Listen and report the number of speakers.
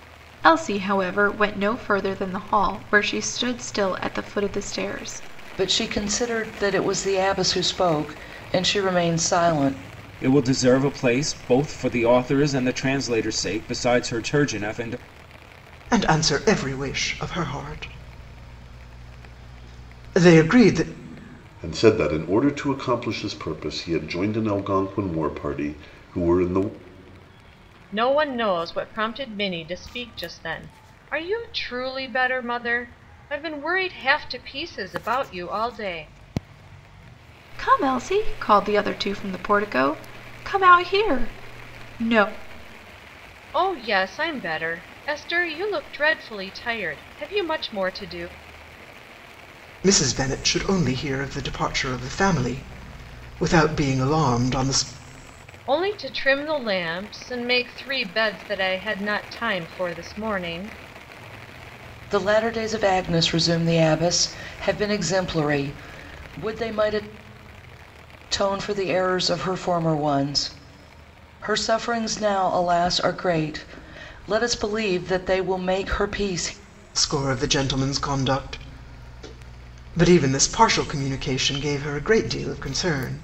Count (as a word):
six